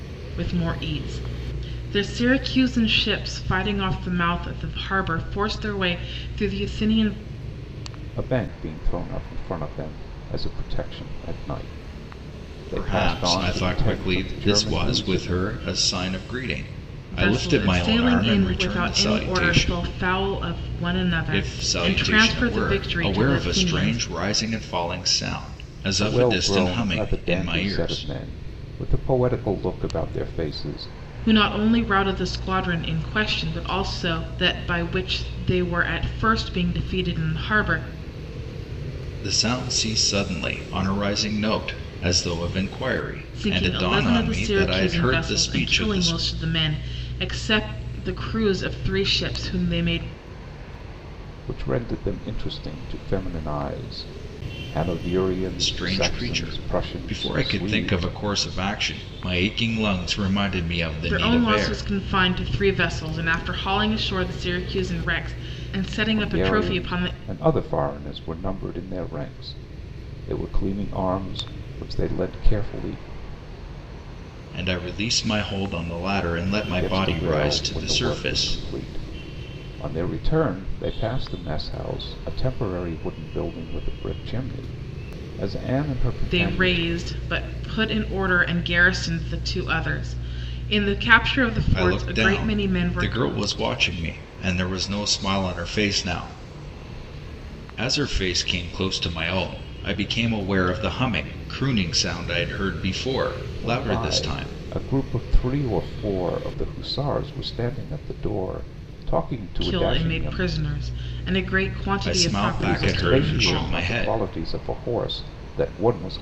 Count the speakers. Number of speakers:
three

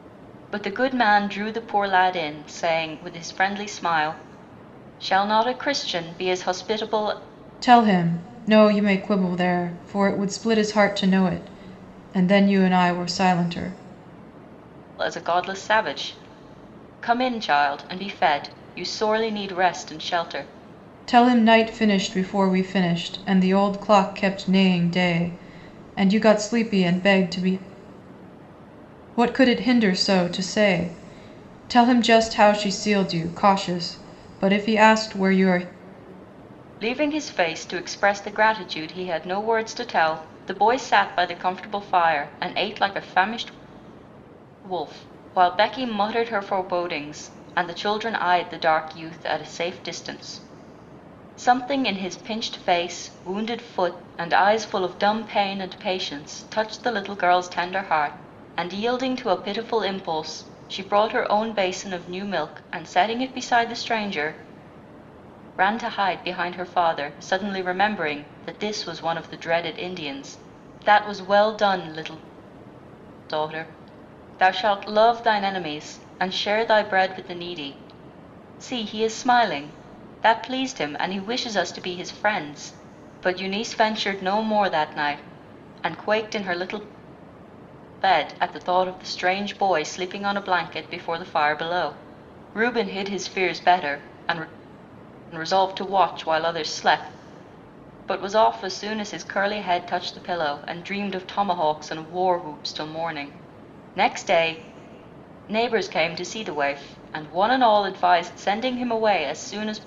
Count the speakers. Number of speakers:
two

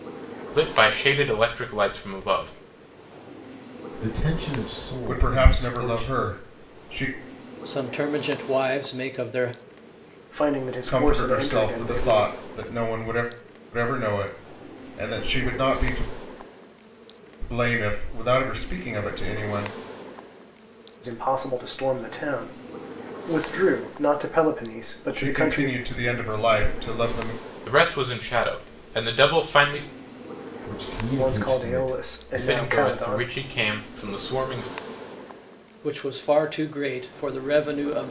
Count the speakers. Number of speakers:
five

